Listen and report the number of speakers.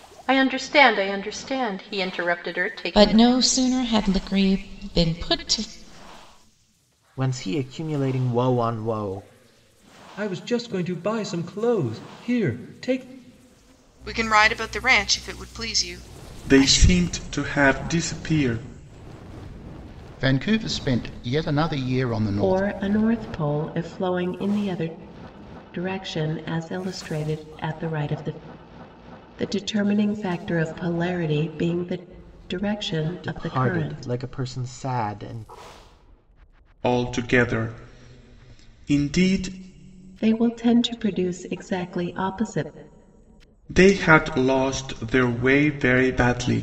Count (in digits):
8